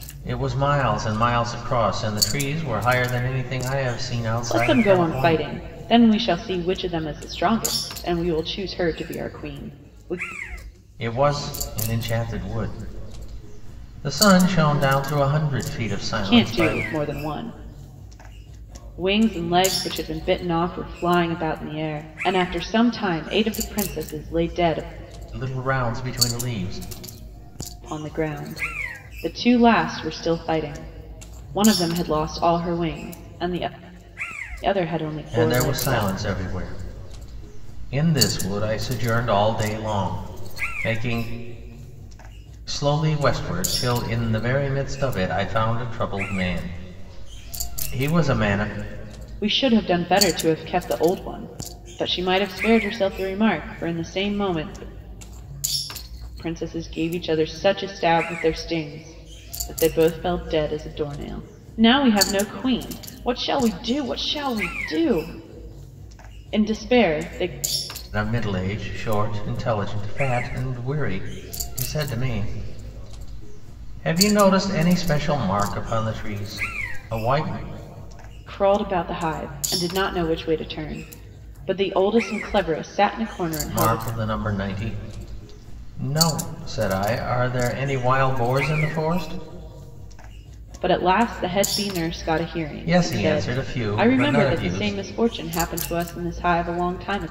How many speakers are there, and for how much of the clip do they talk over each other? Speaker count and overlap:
2, about 5%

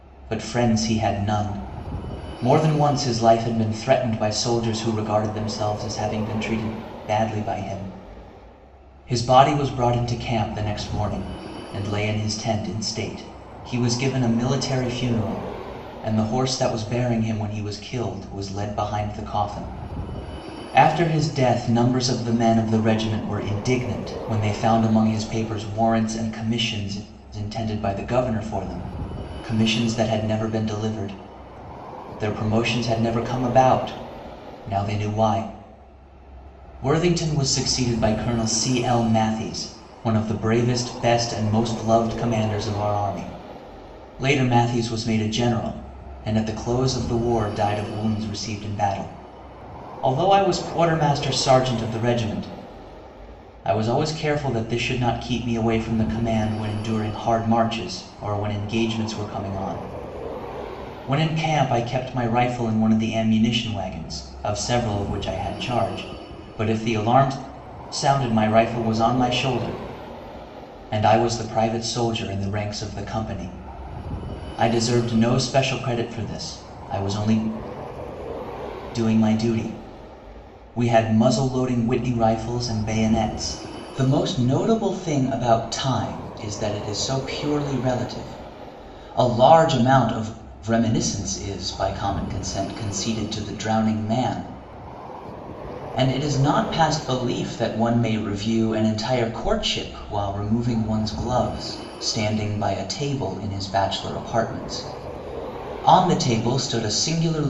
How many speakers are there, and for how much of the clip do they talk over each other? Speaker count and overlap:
1, no overlap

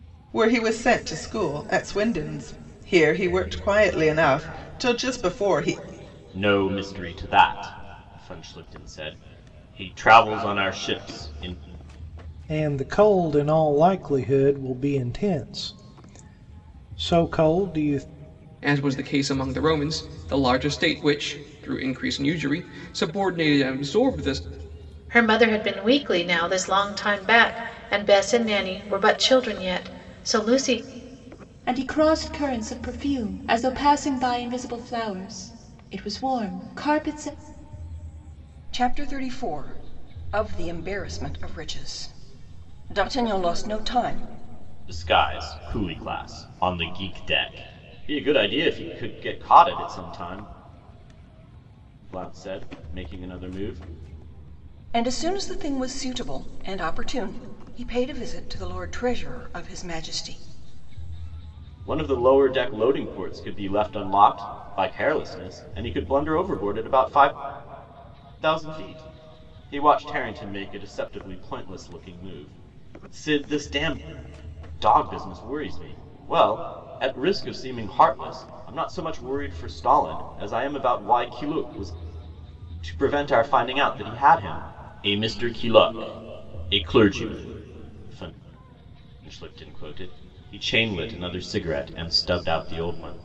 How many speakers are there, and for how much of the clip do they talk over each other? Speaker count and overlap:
7, no overlap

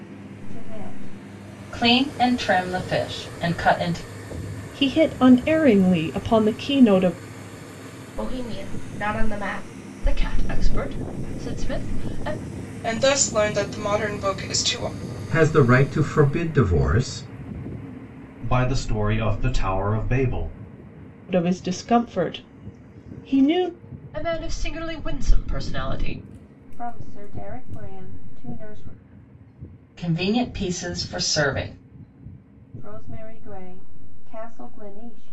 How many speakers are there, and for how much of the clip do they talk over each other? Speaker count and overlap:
8, no overlap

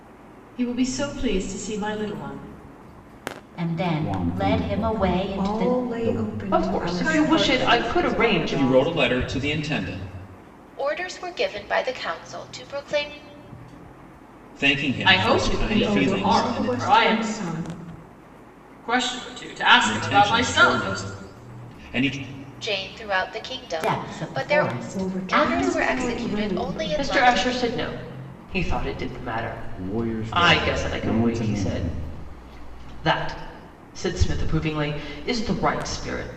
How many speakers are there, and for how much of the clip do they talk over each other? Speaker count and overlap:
8, about 39%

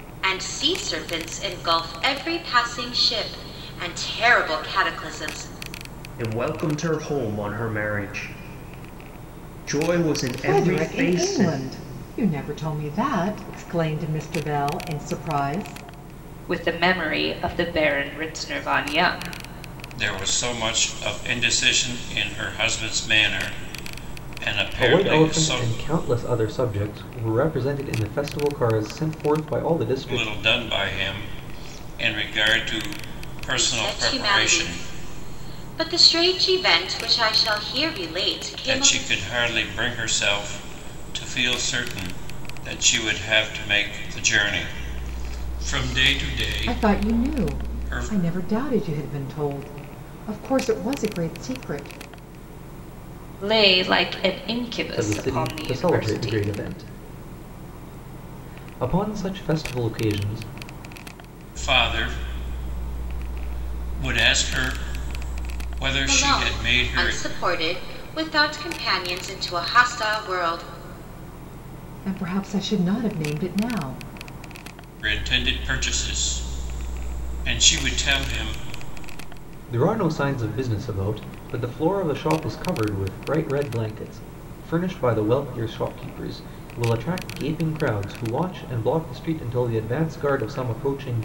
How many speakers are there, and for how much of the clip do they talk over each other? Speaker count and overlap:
6, about 9%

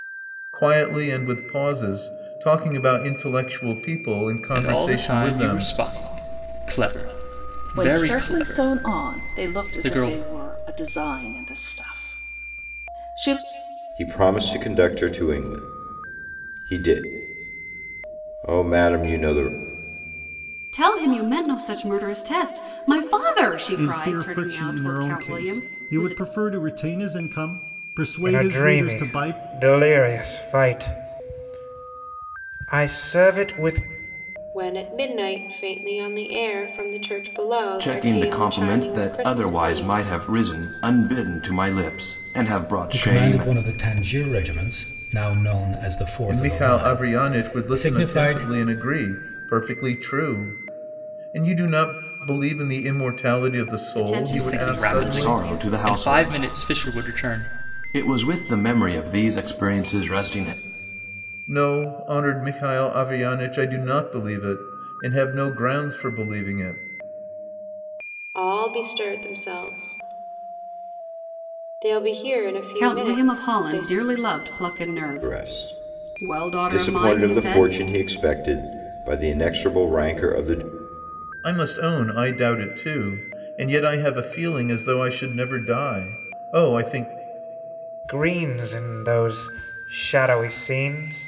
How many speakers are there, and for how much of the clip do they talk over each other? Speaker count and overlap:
10, about 22%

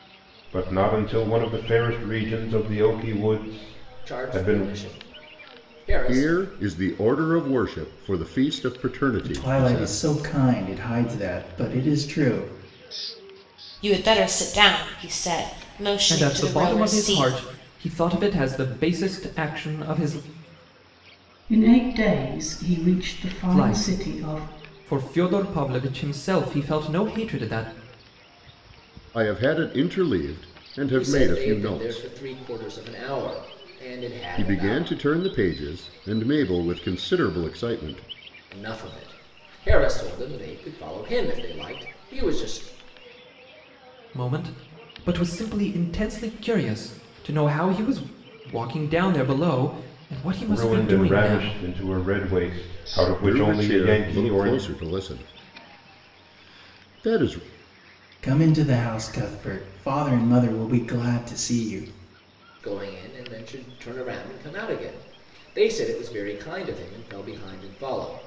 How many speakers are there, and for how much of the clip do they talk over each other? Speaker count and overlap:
7, about 13%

